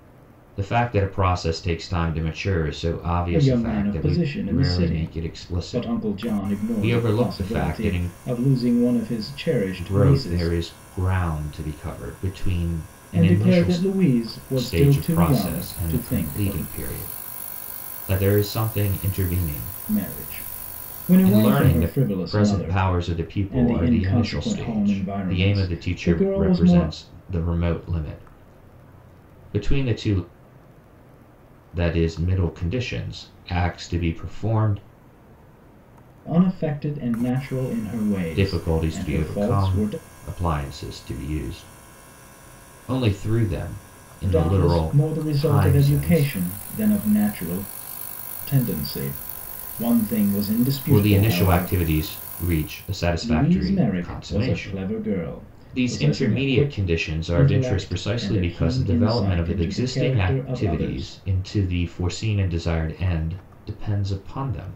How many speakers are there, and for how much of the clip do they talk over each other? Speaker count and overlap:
2, about 39%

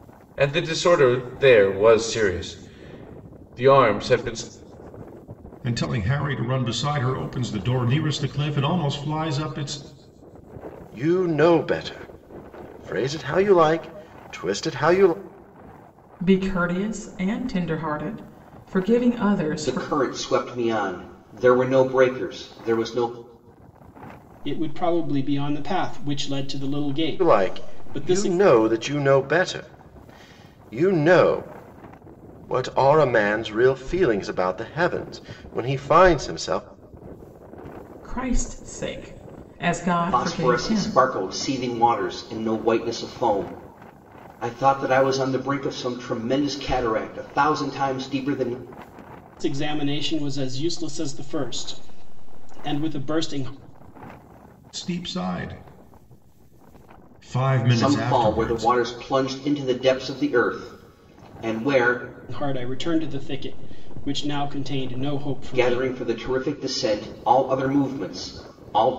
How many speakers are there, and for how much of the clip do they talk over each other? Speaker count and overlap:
6, about 5%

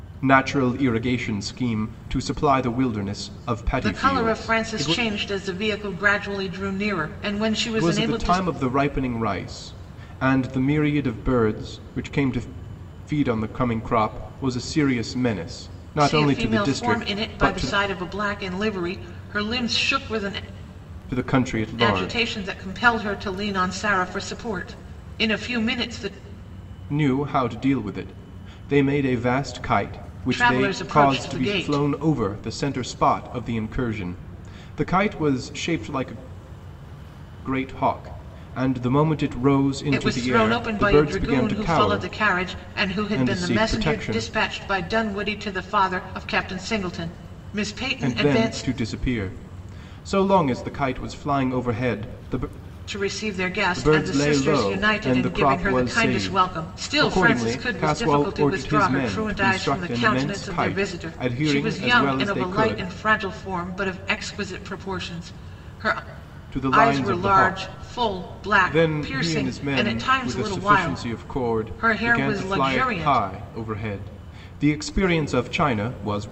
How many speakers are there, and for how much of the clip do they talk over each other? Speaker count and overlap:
2, about 31%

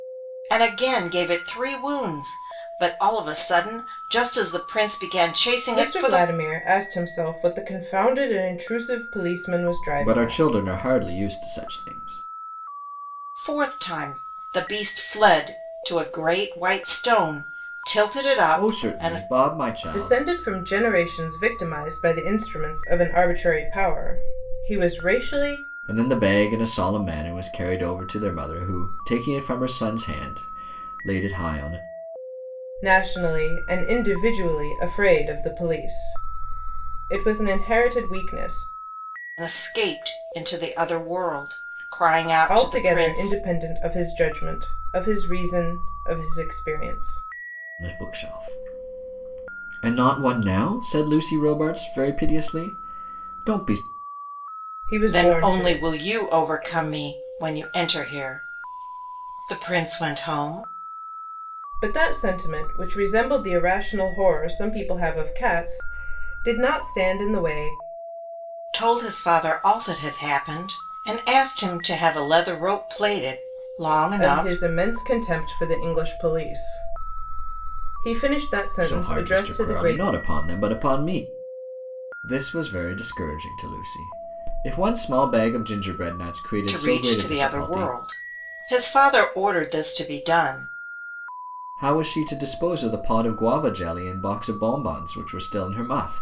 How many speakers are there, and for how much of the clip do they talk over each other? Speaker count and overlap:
3, about 7%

